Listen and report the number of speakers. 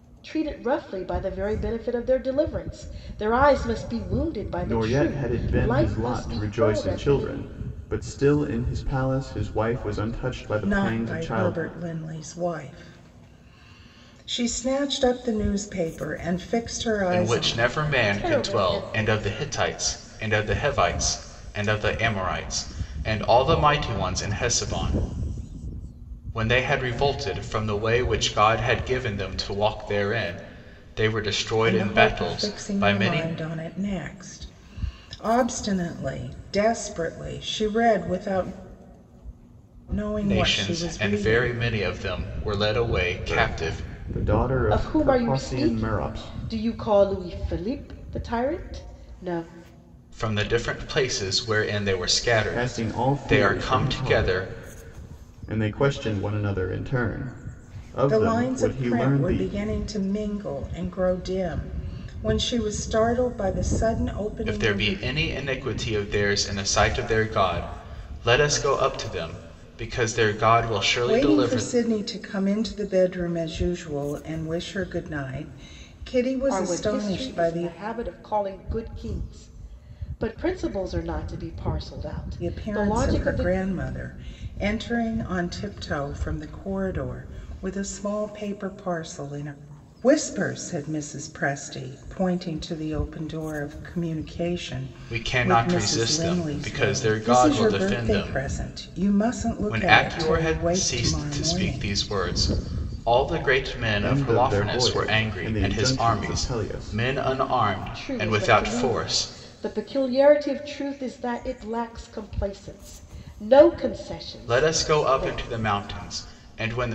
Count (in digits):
4